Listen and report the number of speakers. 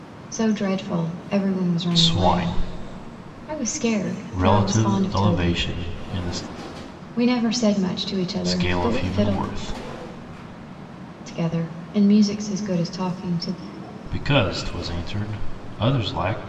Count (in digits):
2